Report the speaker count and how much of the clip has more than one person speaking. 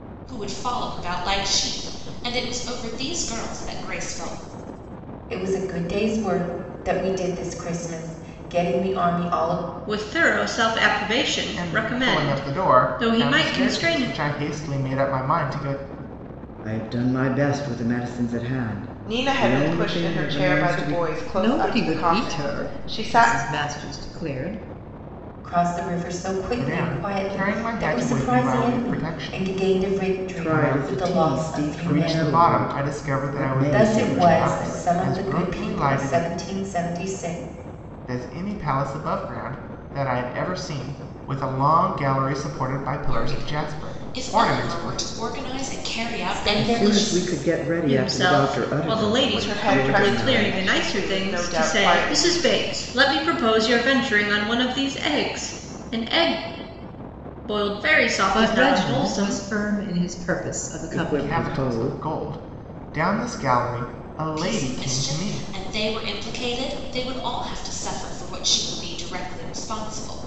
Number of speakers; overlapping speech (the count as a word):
seven, about 39%